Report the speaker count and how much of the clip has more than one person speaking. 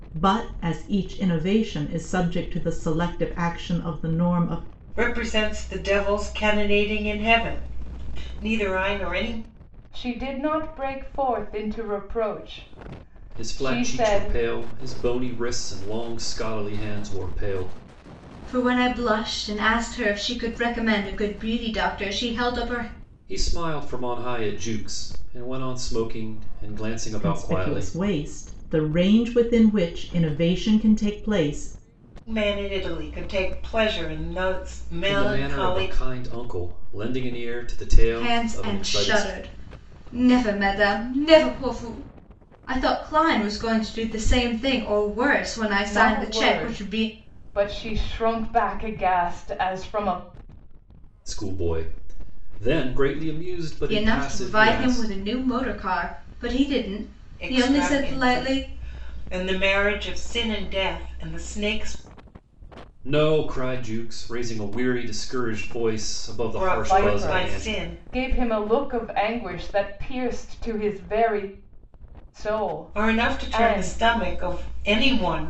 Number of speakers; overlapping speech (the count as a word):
five, about 13%